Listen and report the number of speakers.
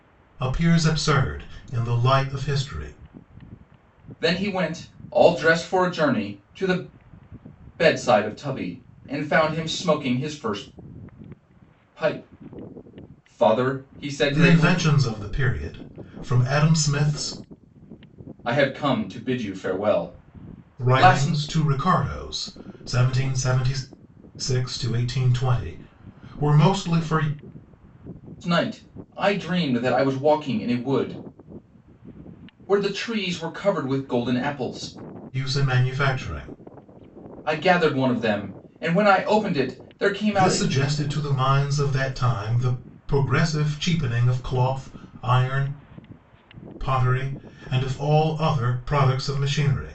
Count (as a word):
two